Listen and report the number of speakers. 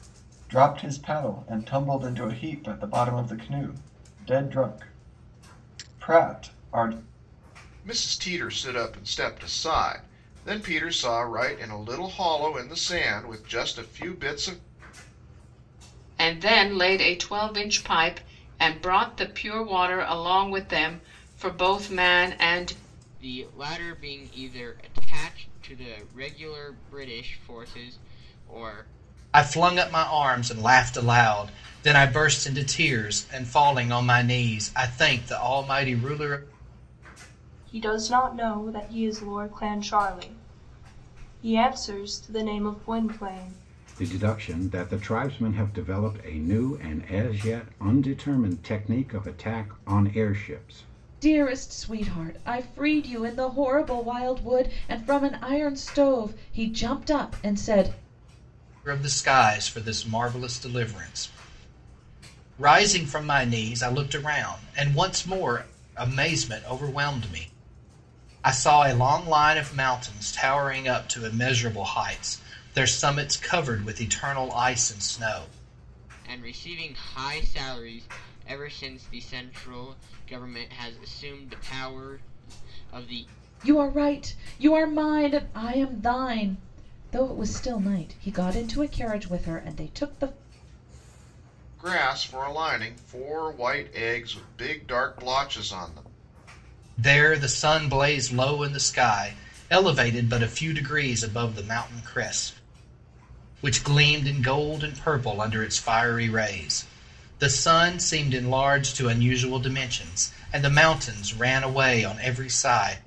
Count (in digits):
8